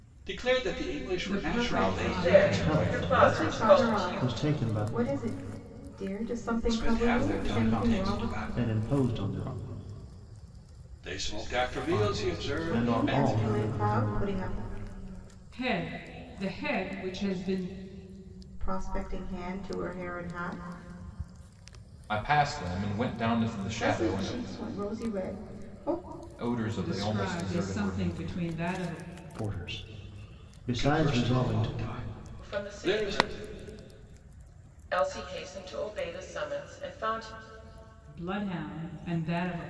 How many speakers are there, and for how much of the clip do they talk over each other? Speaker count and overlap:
6, about 30%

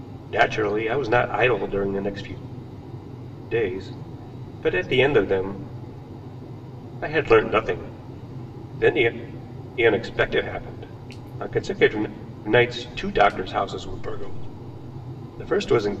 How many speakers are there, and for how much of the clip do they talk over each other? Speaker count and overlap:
1, no overlap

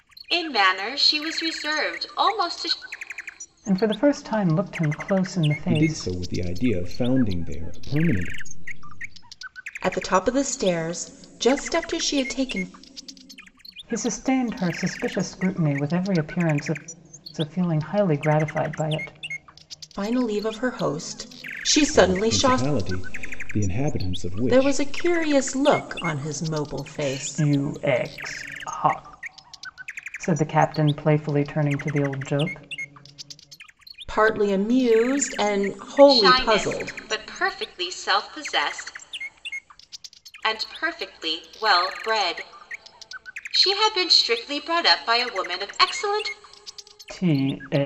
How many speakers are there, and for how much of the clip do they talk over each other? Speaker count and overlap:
4, about 6%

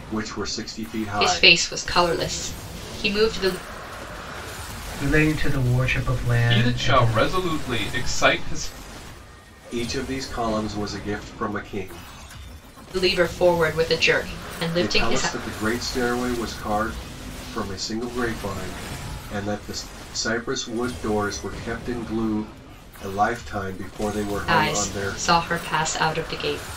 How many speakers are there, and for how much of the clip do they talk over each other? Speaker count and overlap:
4, about 10%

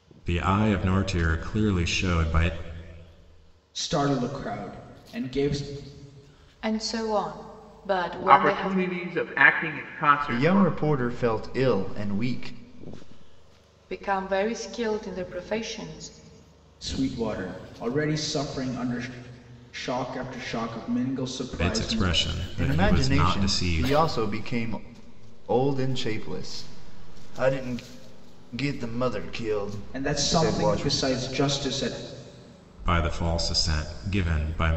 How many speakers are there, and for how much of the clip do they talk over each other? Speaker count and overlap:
5, about 12%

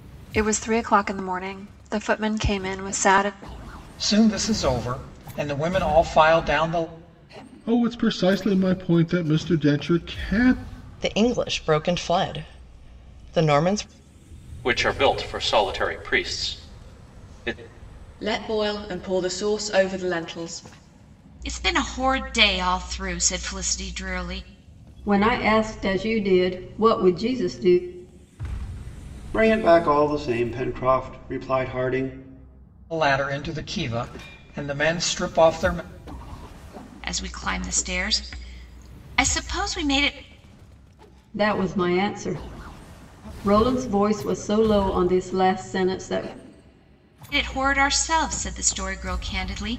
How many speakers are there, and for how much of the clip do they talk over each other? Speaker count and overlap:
9, no overlap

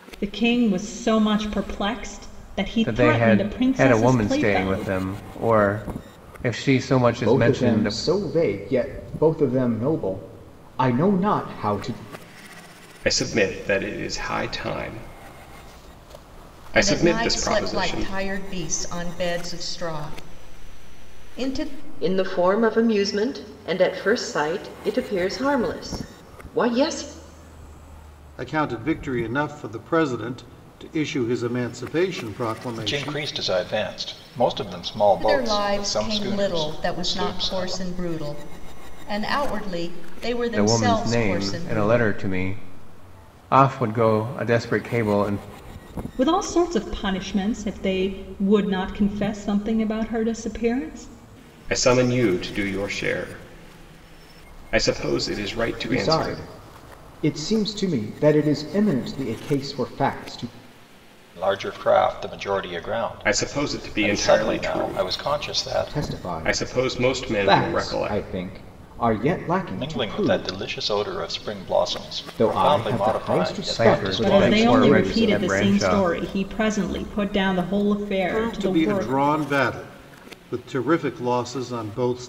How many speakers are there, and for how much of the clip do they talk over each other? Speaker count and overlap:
8, about 25%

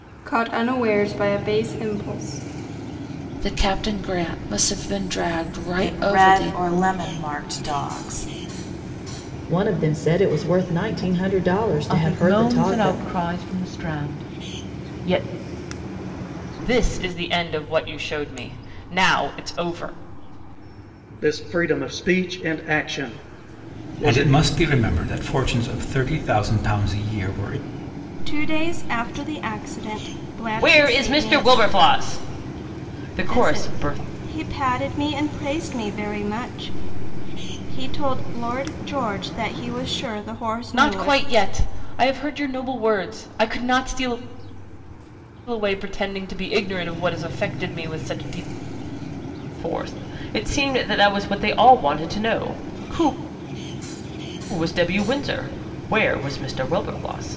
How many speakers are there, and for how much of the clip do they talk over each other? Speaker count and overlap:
10, about 8%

